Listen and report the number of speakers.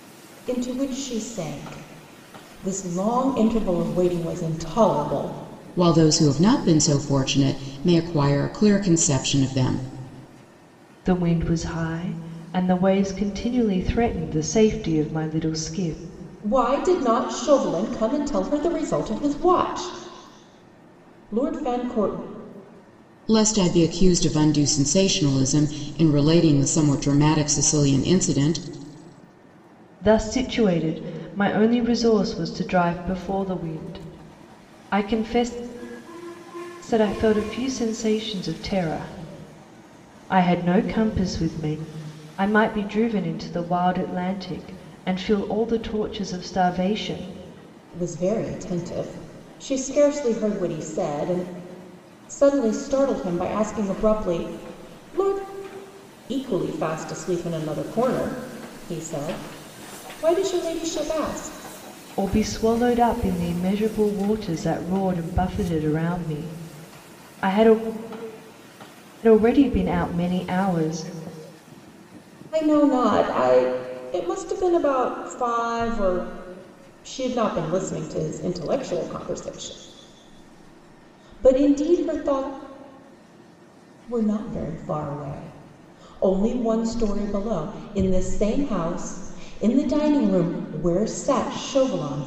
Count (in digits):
3